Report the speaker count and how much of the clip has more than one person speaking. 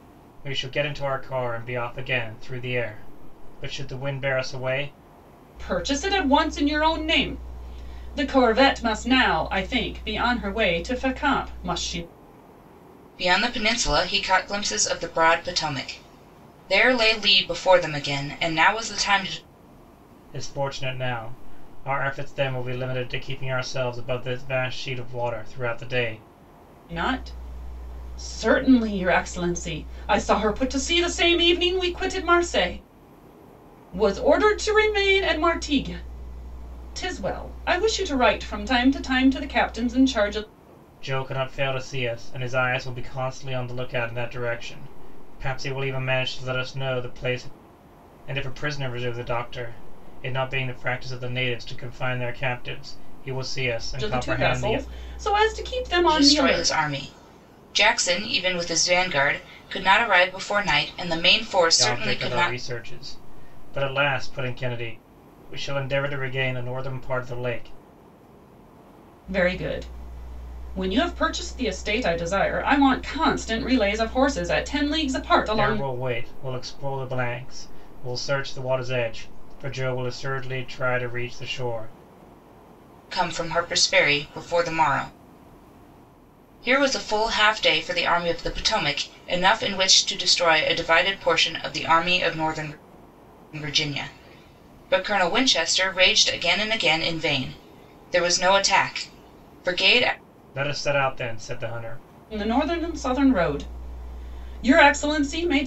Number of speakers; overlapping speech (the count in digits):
3, about 3%